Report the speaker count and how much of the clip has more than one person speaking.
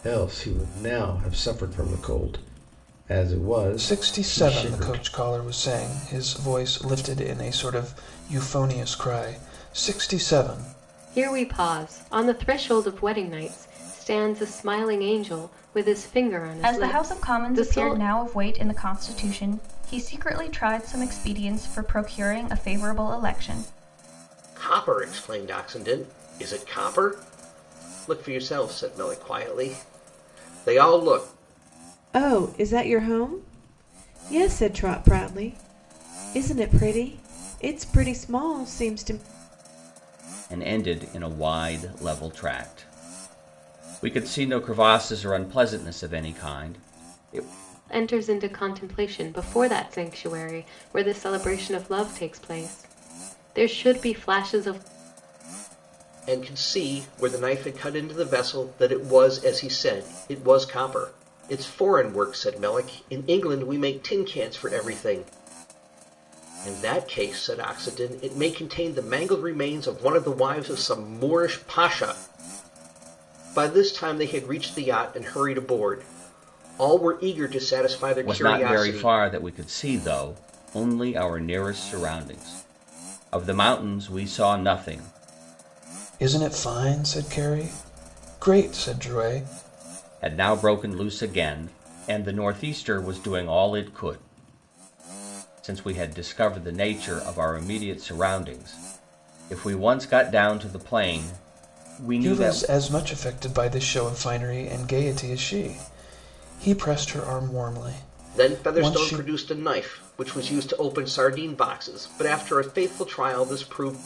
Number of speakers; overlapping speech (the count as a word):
seven, about 4%